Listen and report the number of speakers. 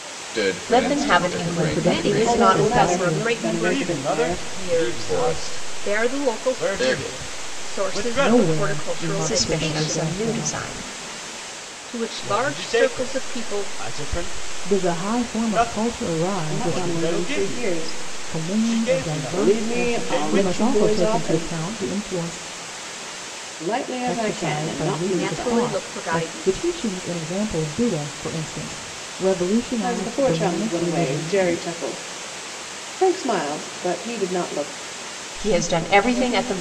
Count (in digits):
6